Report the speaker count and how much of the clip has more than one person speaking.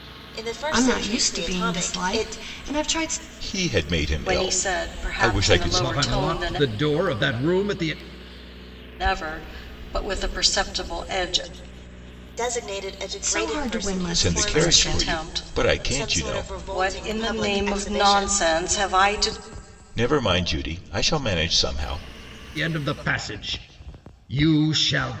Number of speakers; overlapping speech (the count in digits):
5, about 37%